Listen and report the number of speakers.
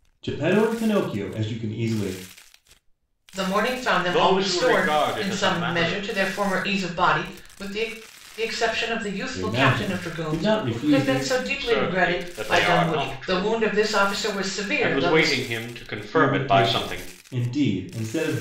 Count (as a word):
three